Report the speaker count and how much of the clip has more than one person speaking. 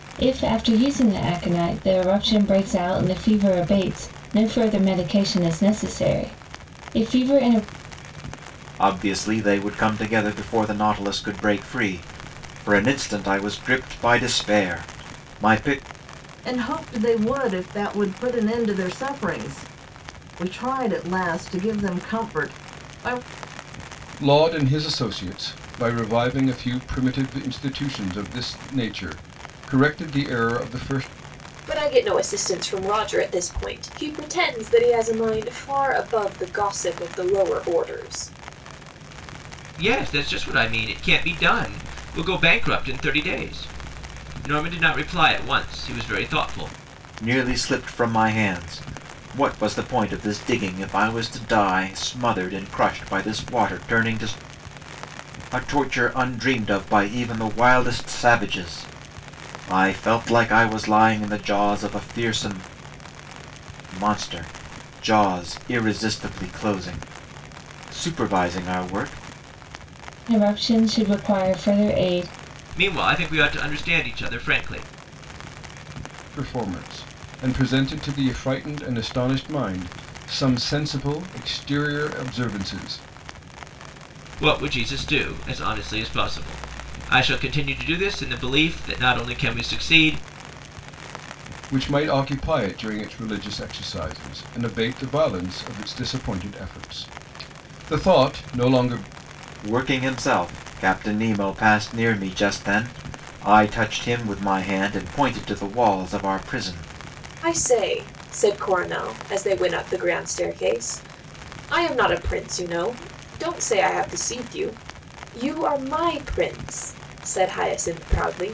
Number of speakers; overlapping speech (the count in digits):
6, no overlap